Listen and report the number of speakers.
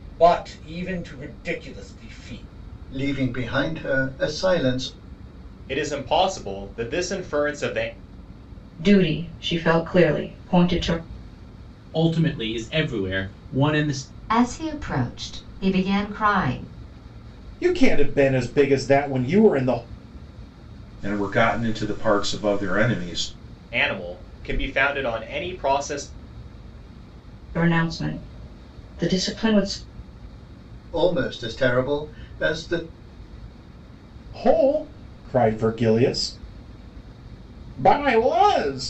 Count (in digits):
8